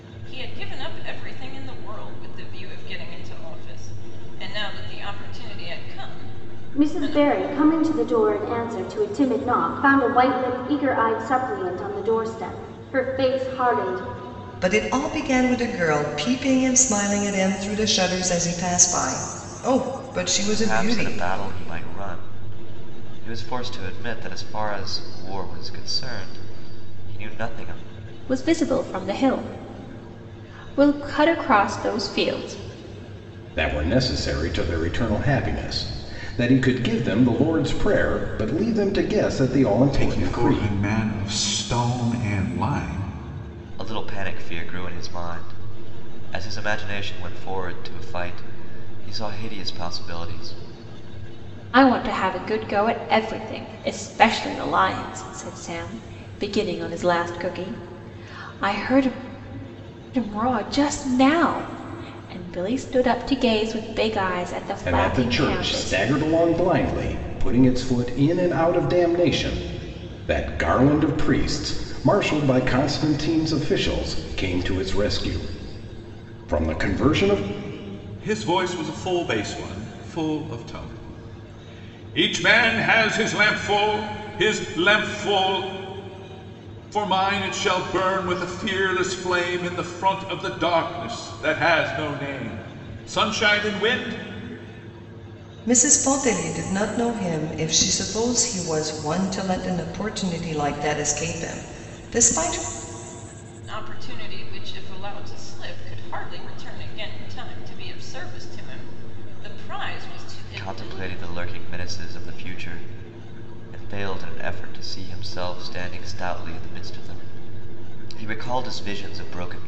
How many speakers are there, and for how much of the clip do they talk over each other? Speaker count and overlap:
seven, about 4%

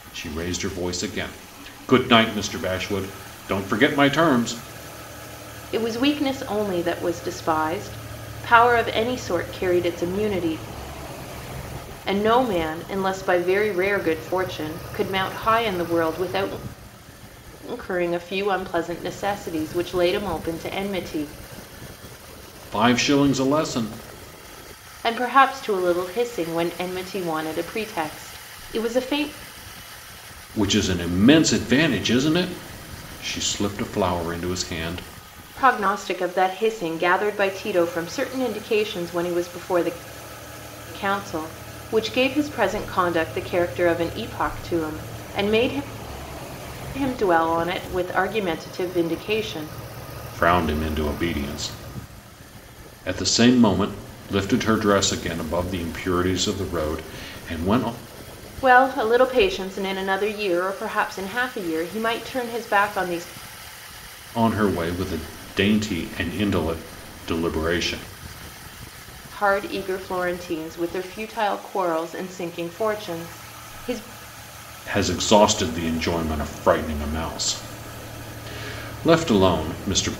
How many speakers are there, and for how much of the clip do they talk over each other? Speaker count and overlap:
two, no overlap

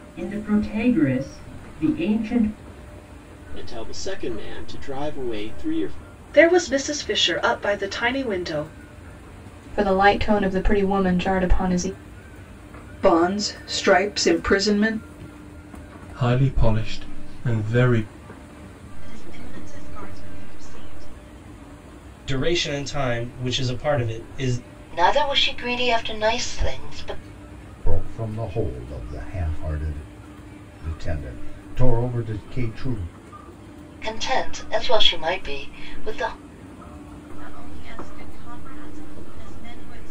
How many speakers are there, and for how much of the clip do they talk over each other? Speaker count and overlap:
ten, no overlap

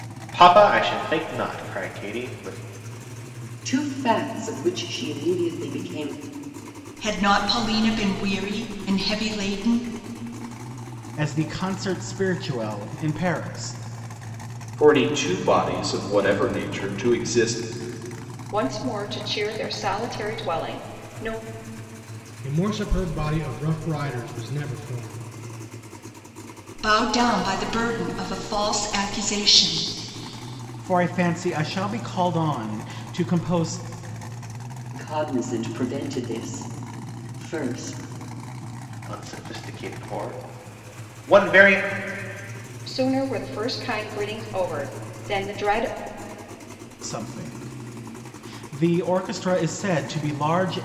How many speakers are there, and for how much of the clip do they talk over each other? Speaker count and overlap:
seven, no overlap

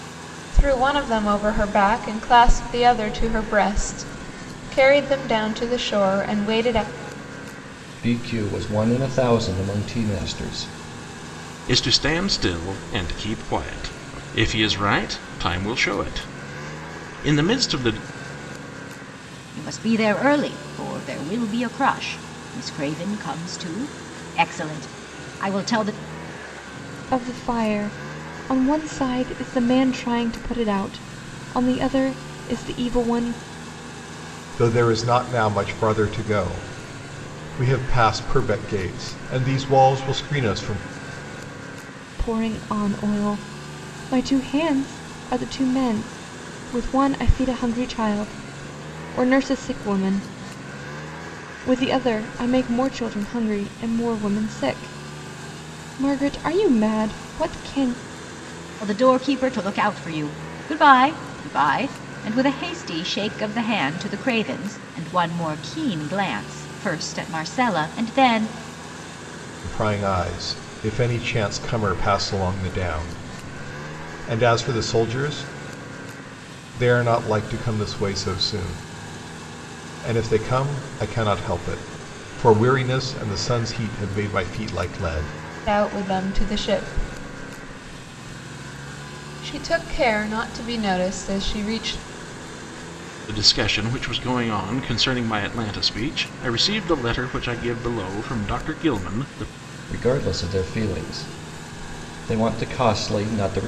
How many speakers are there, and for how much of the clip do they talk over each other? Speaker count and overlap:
six, no overlap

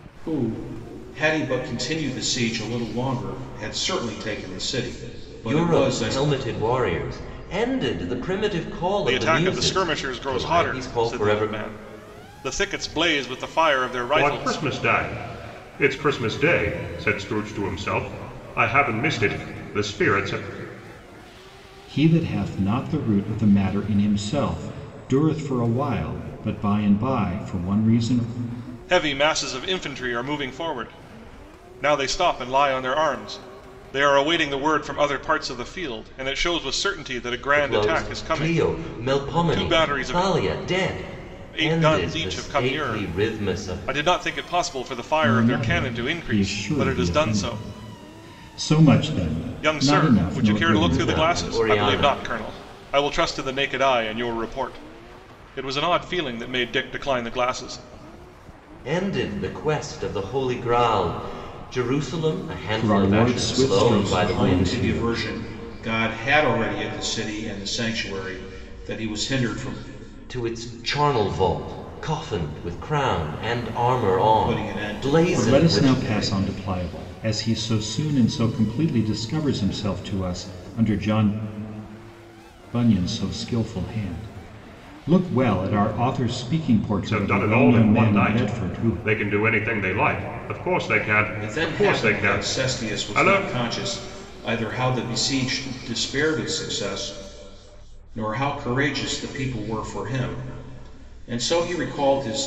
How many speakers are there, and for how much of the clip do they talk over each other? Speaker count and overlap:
five, about 22%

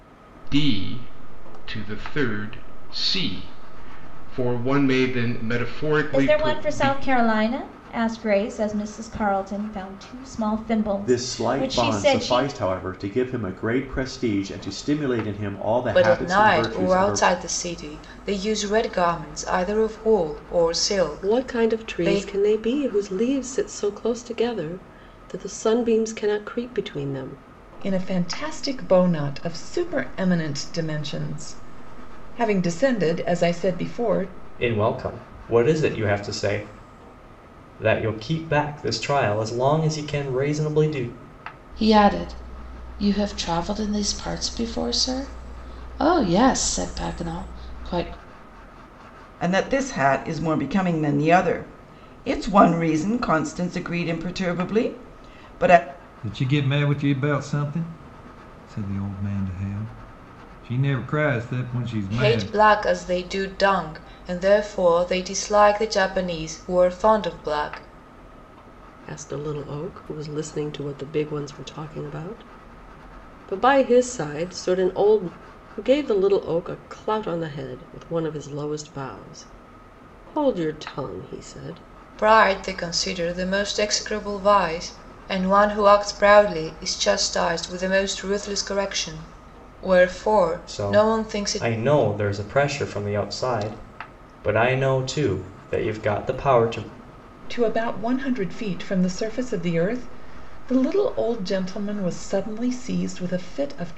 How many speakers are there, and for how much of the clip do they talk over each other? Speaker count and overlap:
ten, about 6%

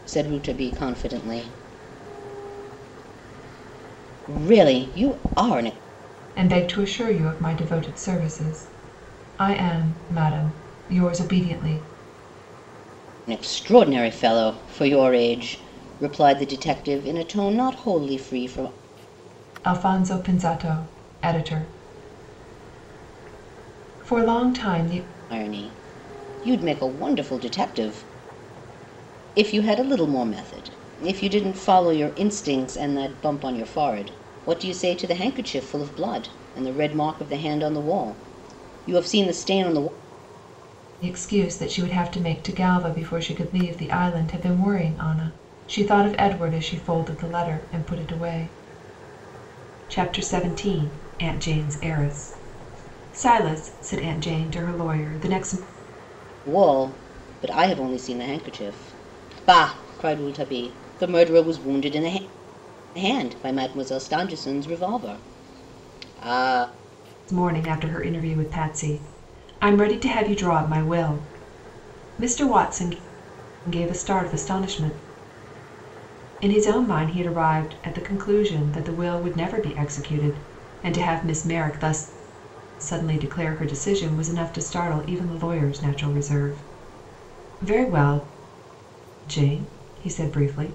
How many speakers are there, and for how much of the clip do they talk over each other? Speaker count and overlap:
two, no overlap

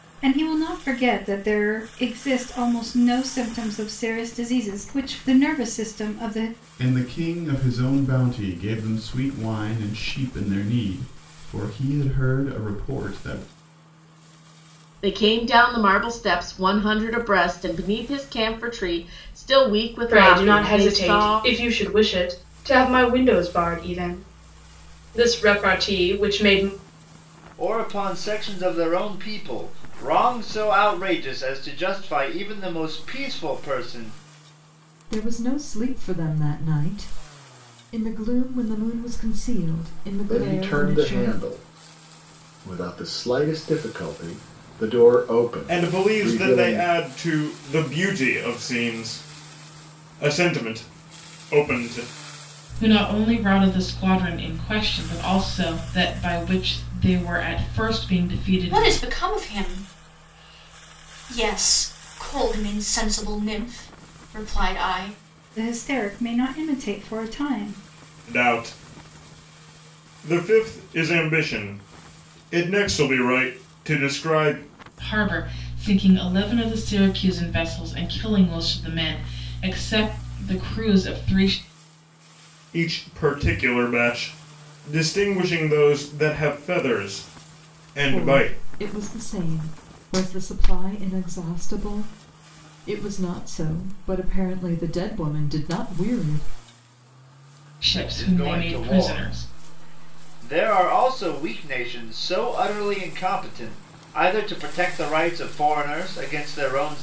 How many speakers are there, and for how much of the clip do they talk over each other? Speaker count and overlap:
ten, about 6%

